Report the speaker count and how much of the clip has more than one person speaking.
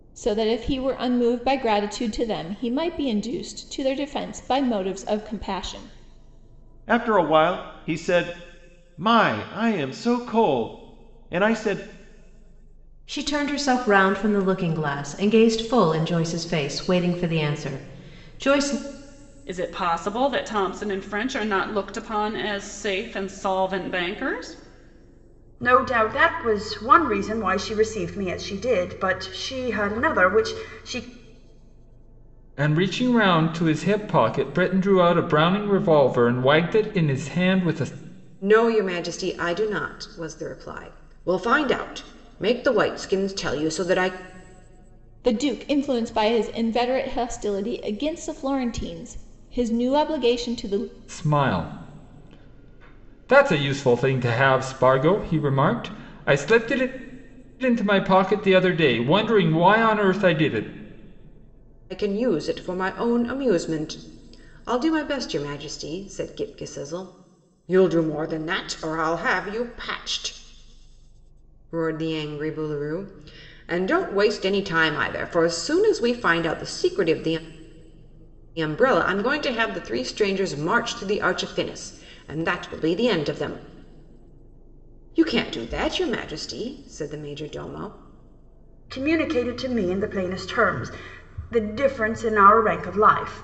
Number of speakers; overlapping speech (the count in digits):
7, no overlap